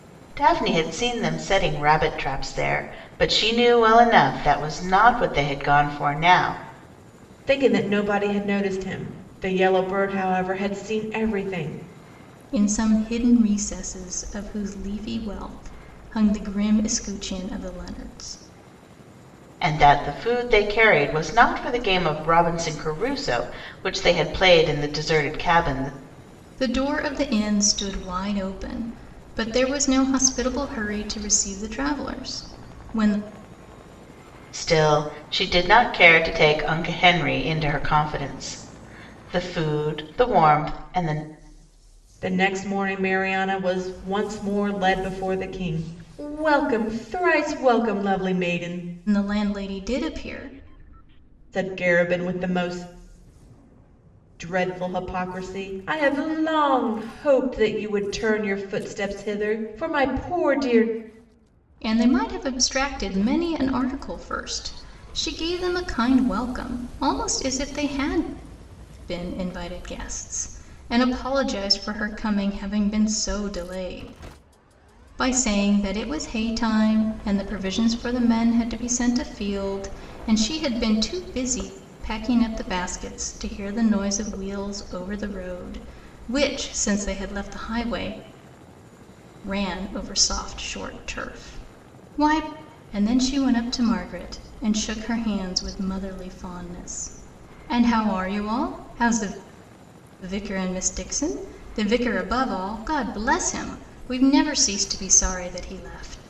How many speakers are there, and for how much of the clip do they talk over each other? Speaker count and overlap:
three, no overlap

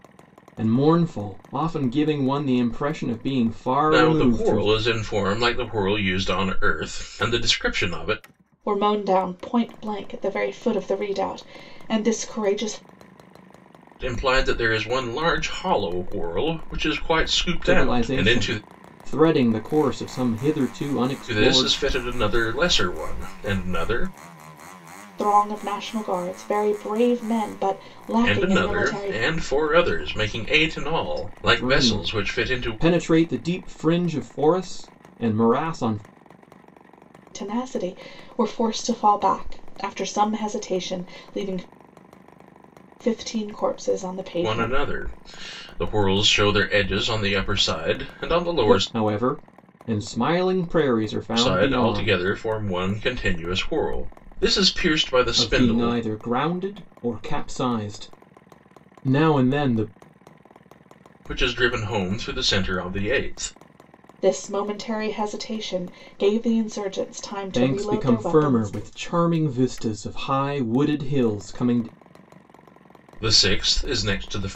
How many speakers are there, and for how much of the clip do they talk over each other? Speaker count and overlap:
three, about 11%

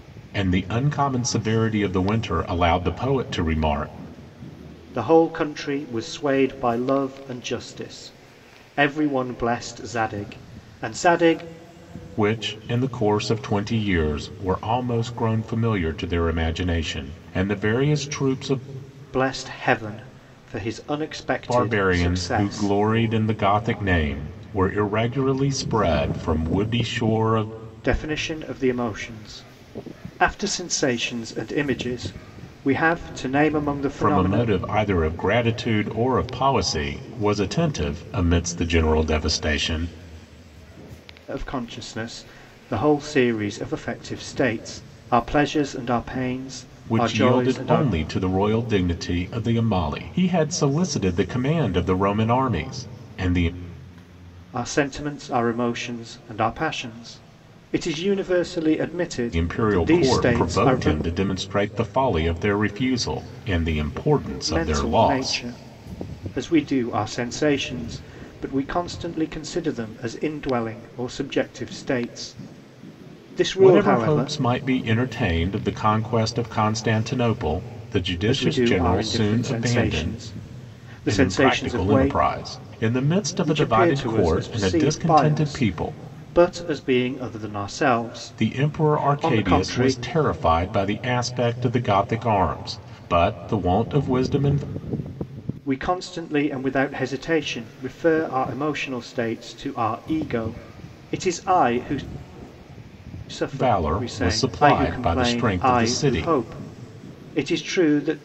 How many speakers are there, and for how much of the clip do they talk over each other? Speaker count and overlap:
two, about 15%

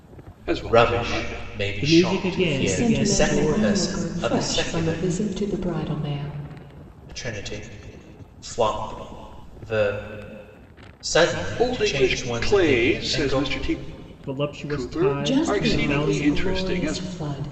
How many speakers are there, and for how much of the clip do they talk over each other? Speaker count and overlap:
four, about 49%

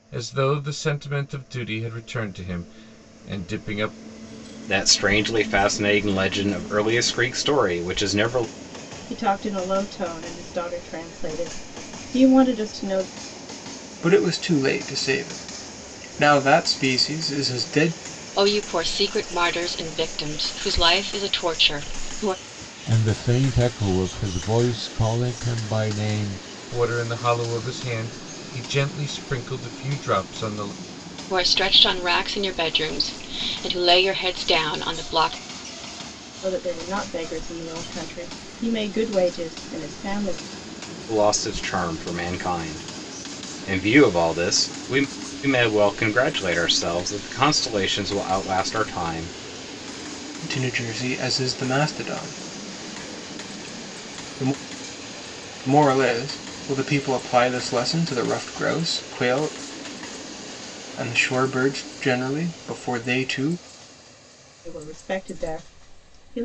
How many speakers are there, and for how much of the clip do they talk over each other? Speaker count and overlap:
six, no overlap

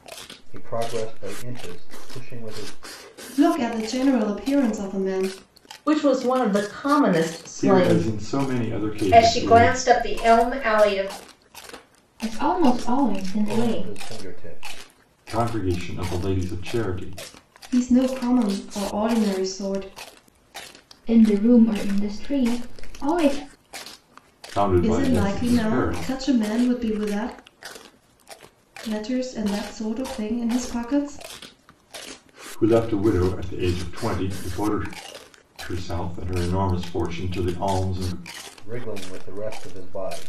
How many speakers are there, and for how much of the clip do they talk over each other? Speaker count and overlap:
six, about 10%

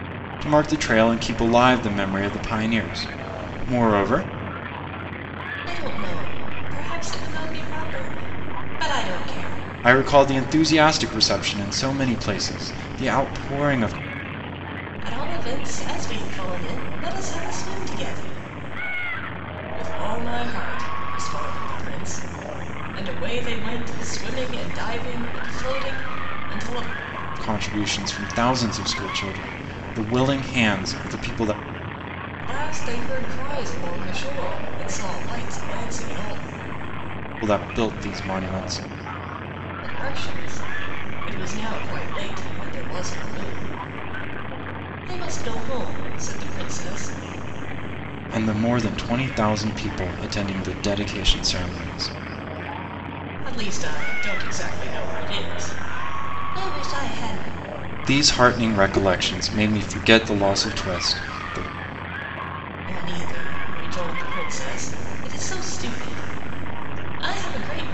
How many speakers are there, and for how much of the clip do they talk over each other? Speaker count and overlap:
two, no overlap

